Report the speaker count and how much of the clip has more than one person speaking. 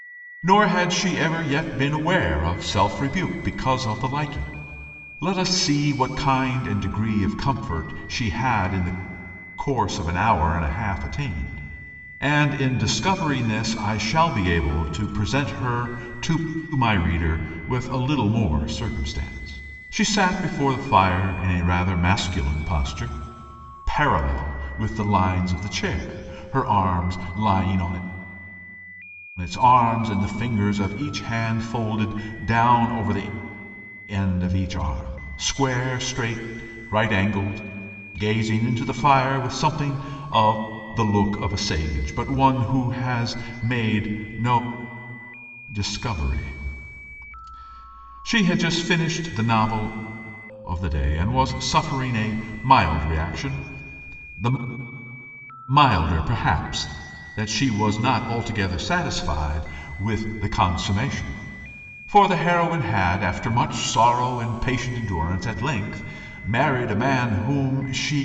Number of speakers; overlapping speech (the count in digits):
1, no overlap